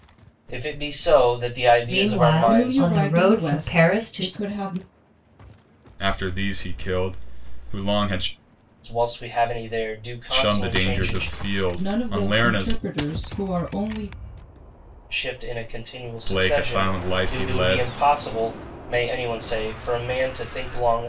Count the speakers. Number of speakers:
4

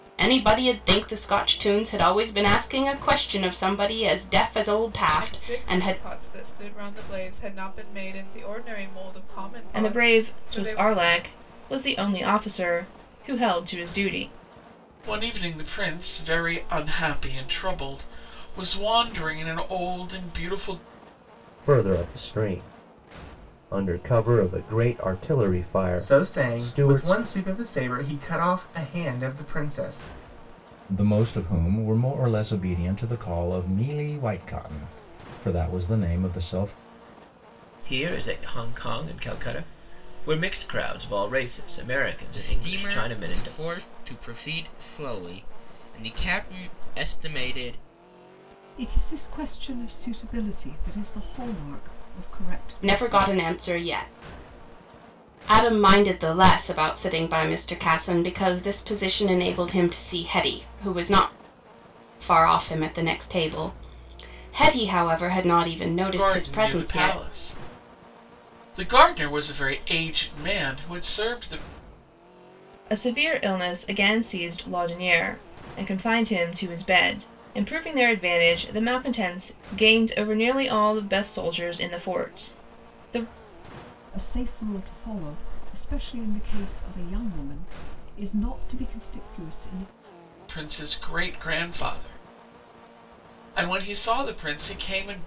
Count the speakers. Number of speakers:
10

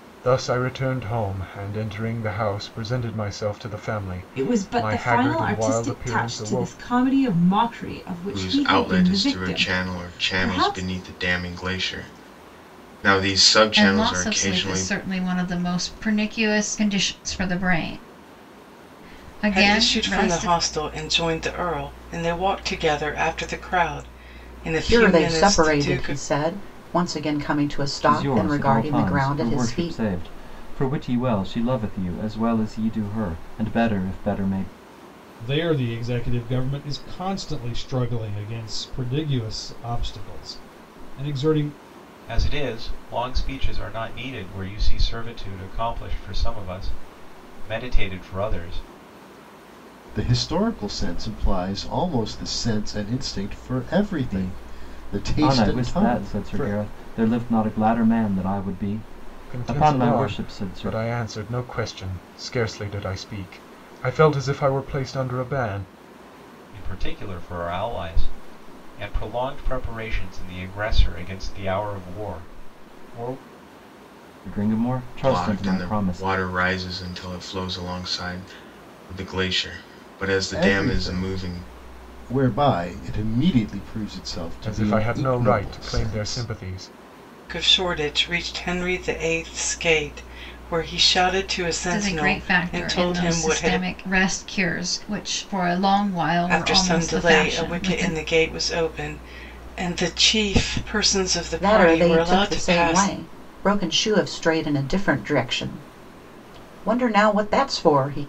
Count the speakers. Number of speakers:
10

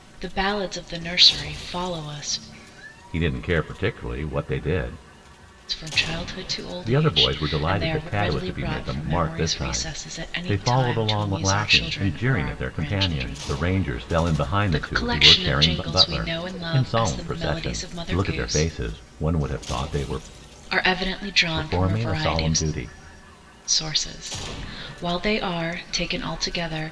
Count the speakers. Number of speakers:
2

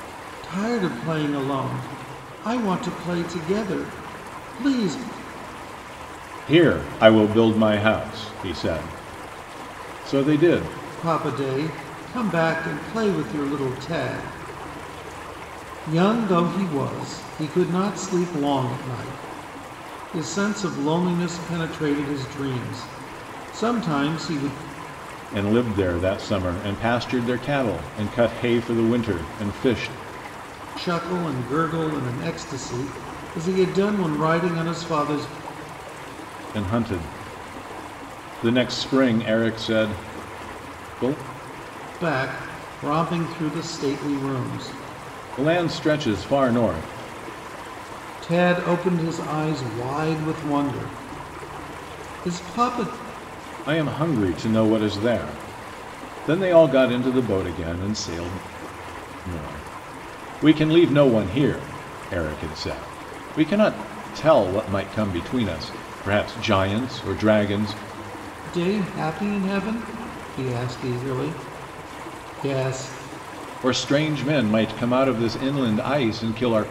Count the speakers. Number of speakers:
2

